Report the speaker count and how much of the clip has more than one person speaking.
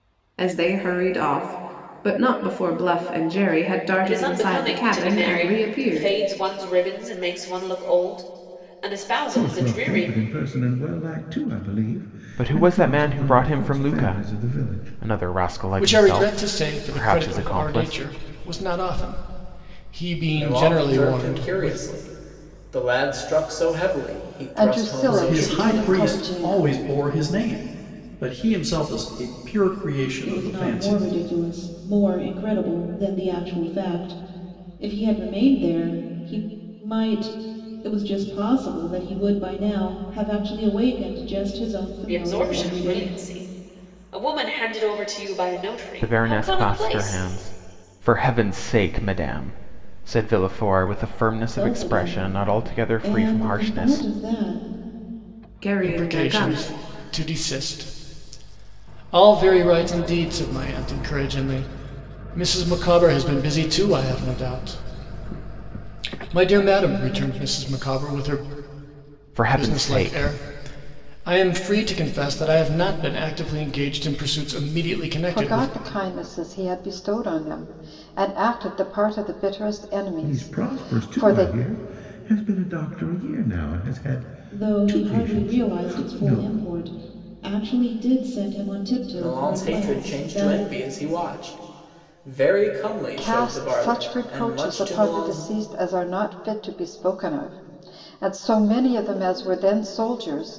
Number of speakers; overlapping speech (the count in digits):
9, about 27%